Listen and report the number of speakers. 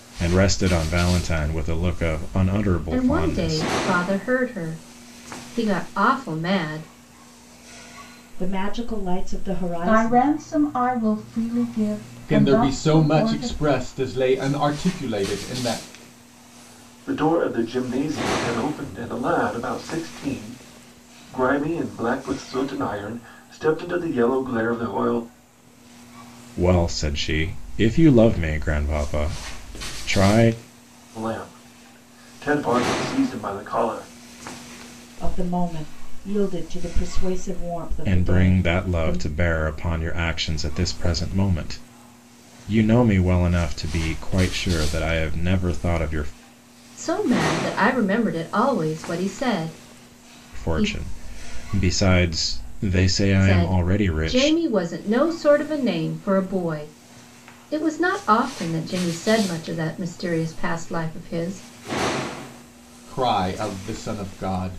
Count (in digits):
6